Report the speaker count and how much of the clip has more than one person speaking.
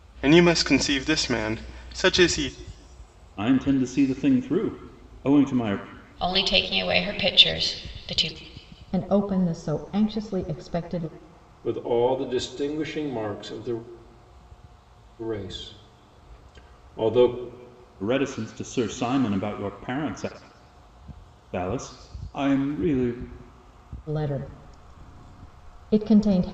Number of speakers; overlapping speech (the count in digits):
5, no overlap